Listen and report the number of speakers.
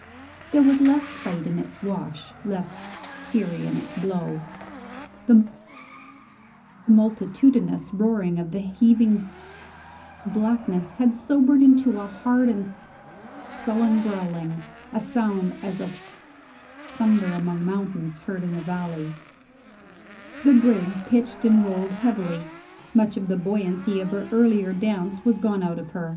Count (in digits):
1